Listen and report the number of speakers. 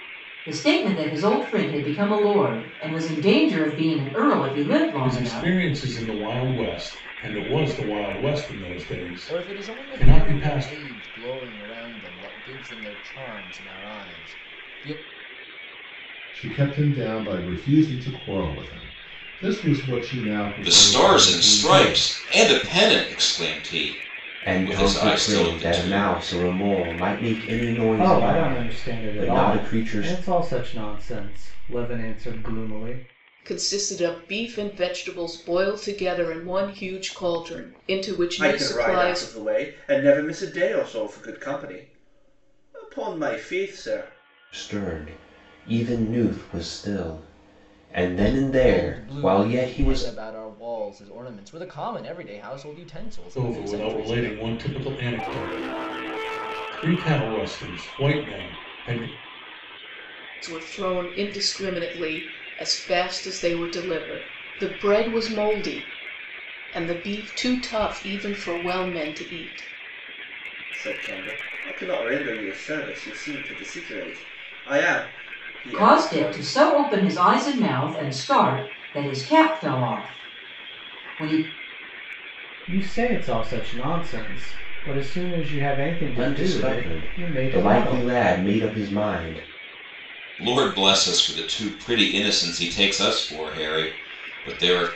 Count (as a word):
nine